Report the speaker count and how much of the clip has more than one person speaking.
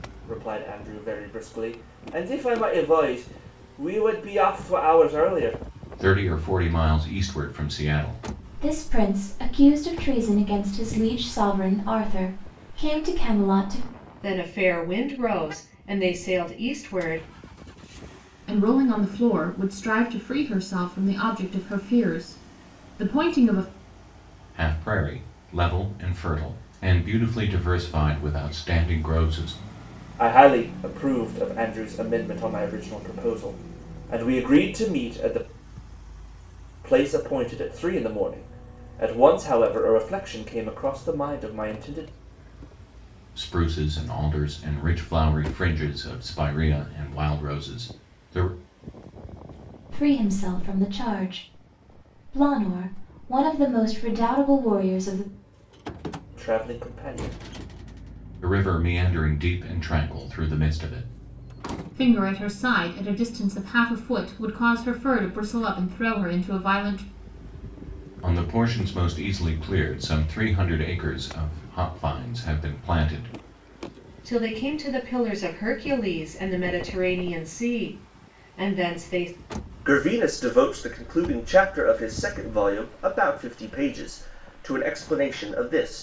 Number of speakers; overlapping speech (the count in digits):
5, no overlap